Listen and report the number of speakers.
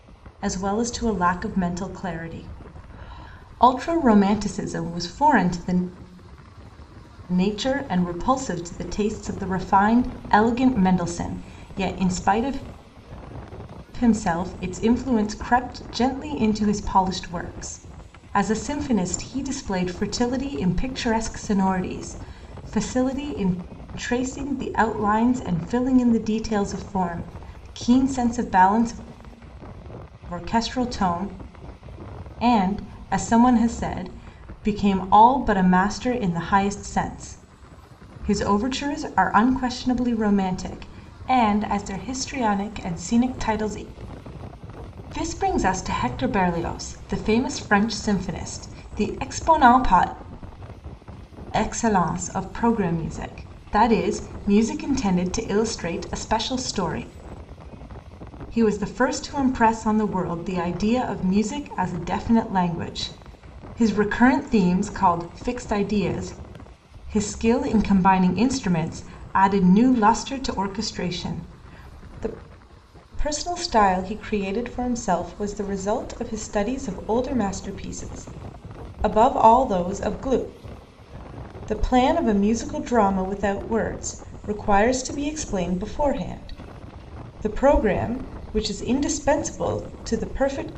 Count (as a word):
one